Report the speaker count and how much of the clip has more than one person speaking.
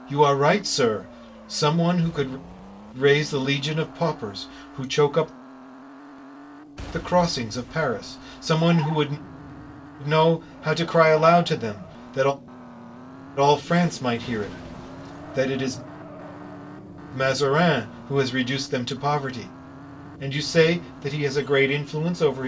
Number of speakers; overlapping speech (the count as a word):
one, no overlap